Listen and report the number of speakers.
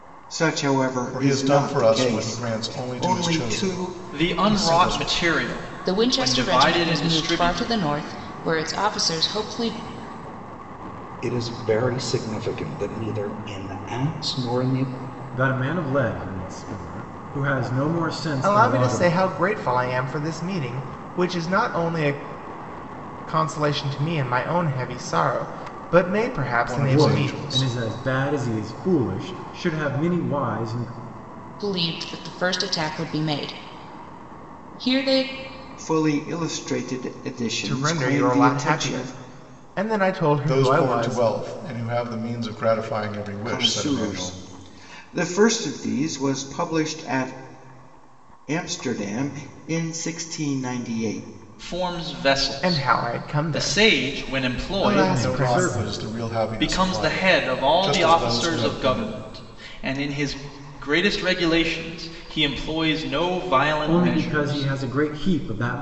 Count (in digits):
7